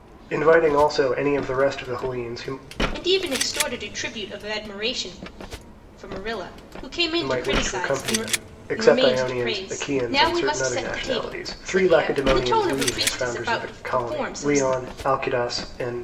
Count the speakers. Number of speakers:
2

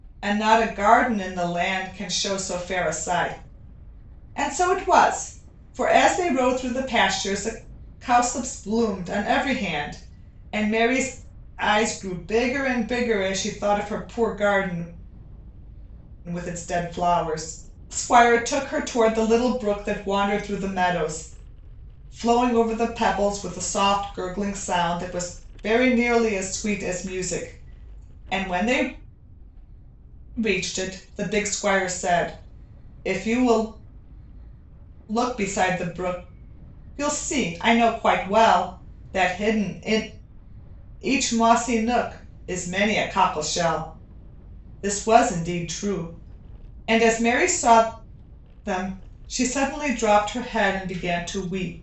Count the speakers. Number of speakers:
1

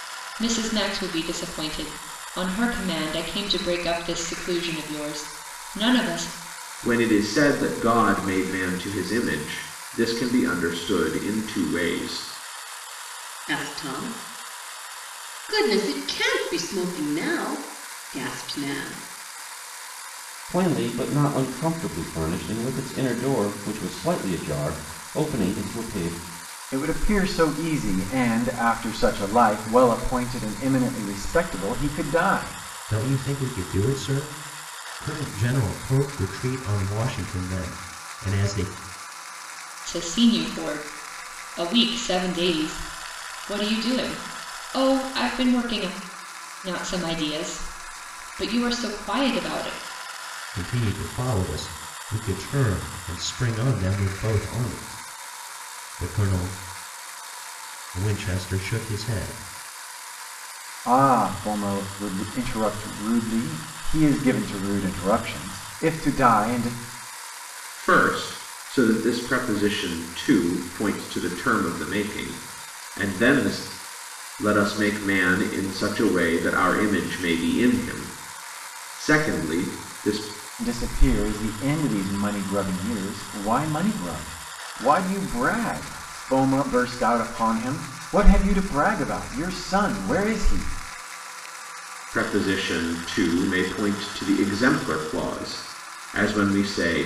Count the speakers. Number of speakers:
6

